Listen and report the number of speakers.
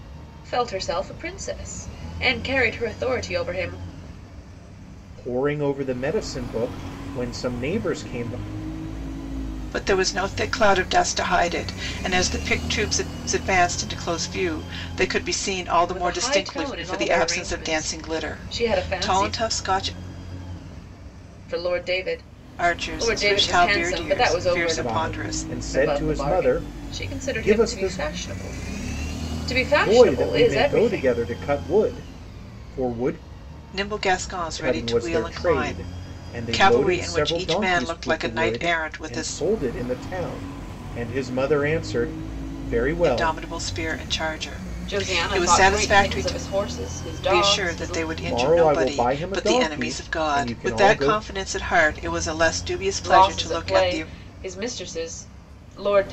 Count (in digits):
3